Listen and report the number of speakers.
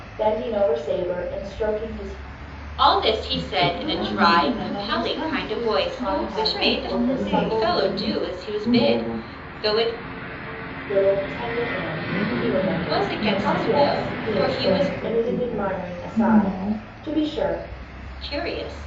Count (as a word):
four